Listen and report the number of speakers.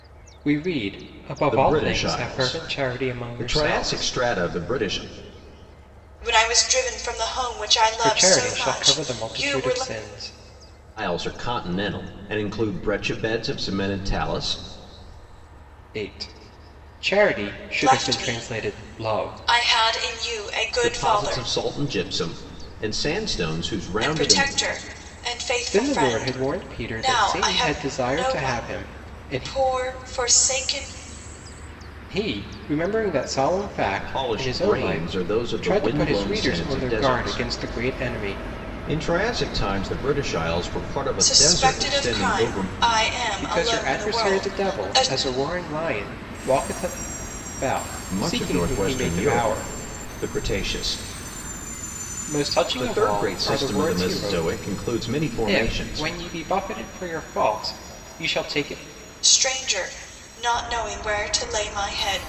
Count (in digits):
3